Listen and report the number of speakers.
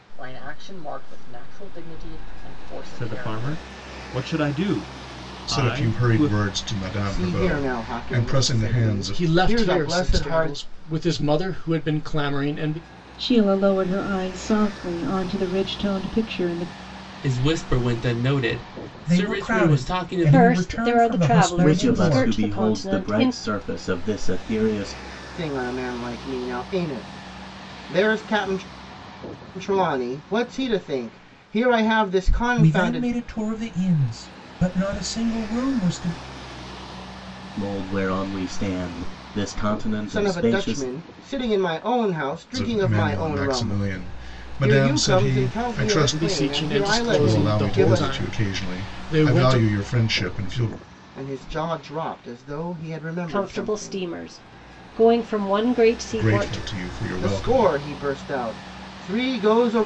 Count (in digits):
10